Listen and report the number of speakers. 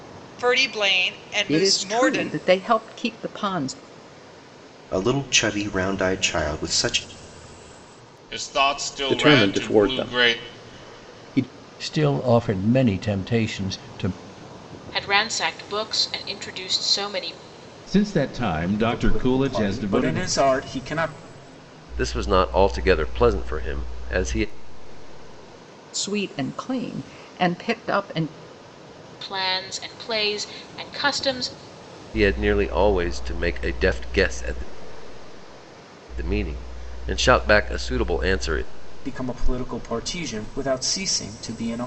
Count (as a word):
ten